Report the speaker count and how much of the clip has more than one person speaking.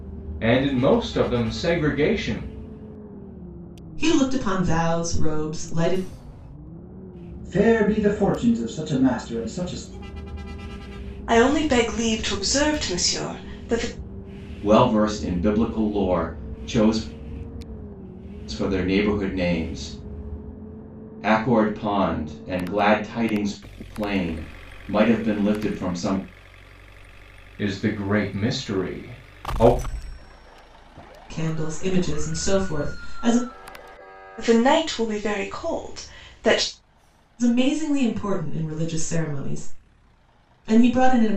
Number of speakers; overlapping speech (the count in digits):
5, no overlap